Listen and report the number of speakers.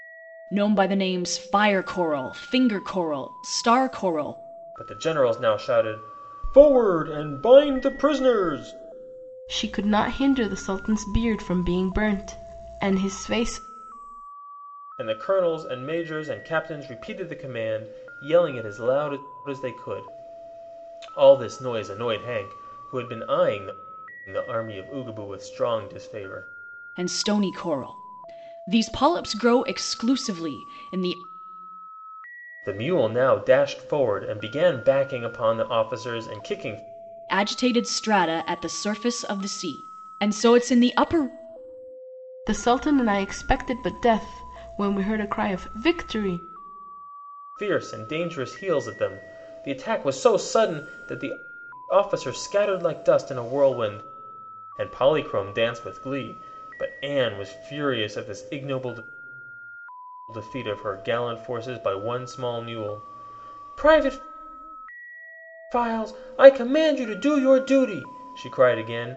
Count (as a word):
three